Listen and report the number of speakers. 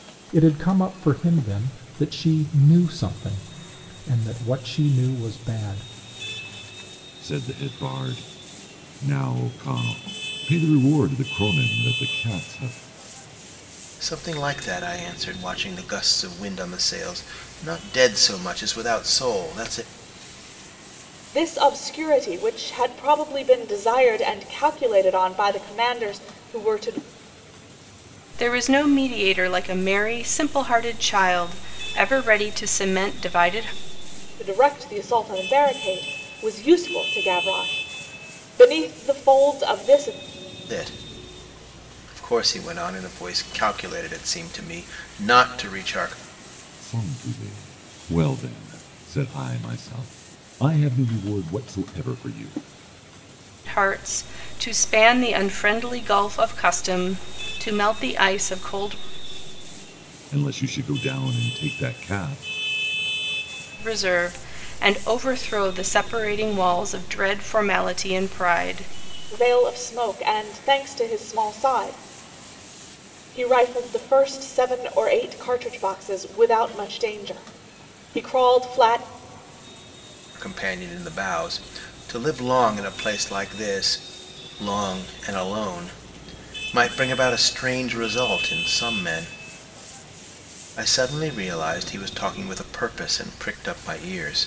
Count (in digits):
5